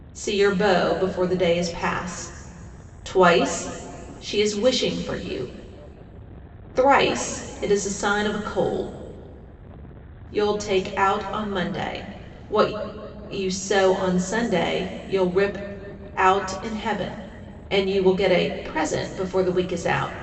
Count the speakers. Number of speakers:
1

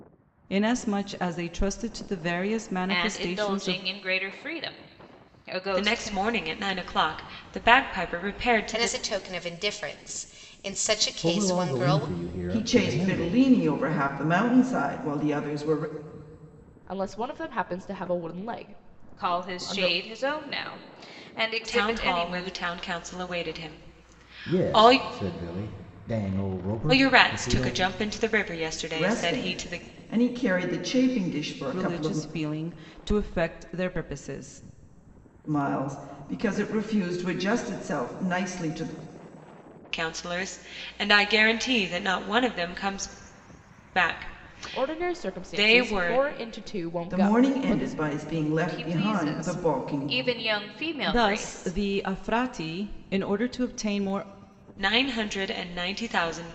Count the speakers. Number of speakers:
7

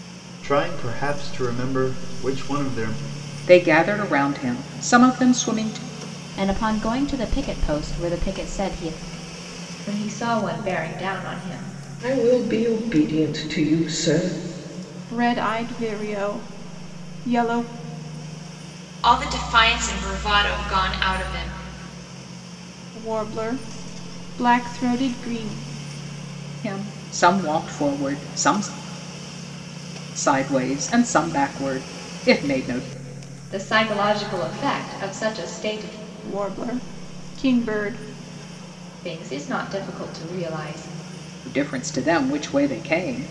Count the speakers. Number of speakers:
7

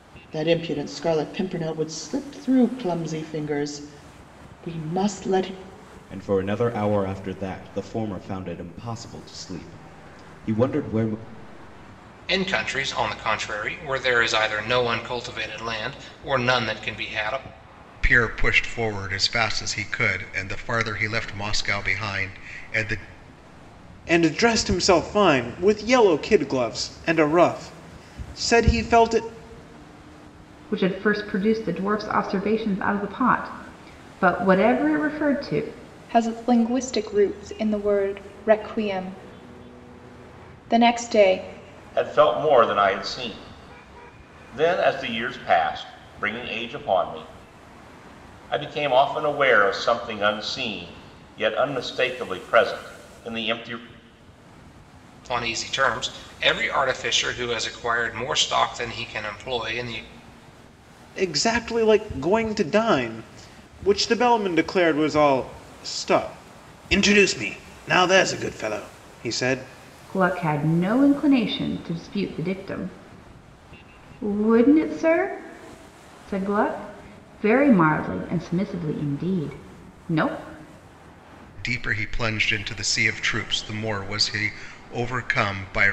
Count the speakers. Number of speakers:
8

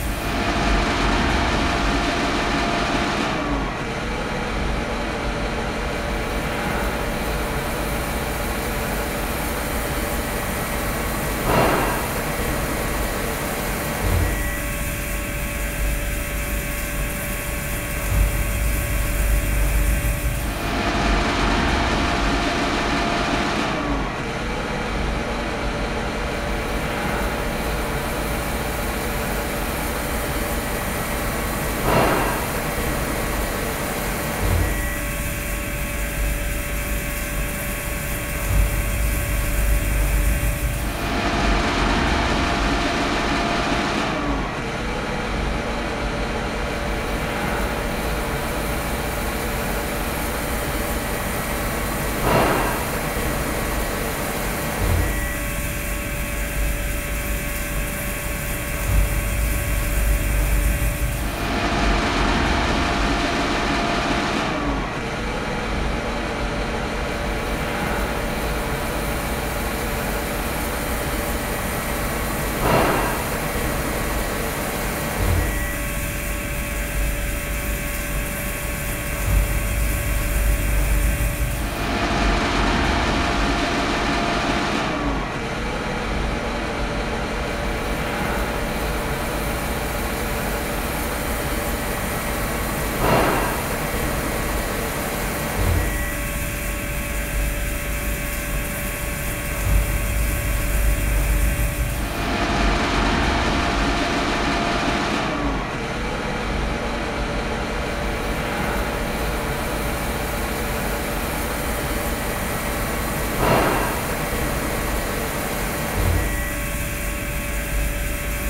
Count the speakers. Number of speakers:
0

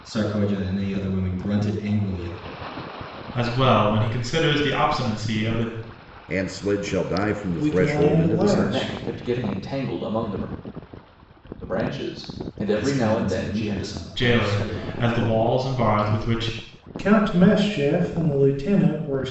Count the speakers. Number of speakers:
5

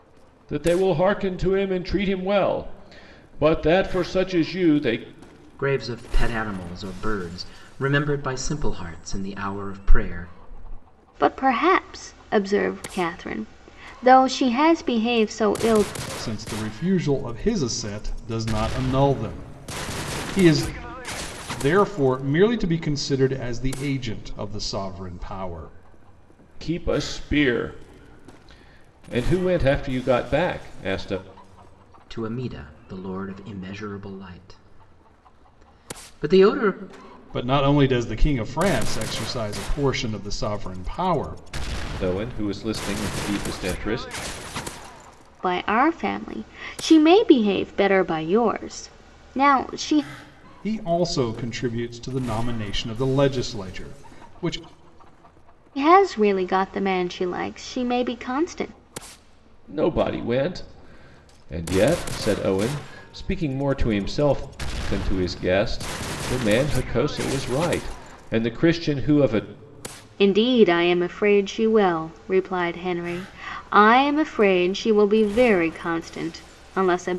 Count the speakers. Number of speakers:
4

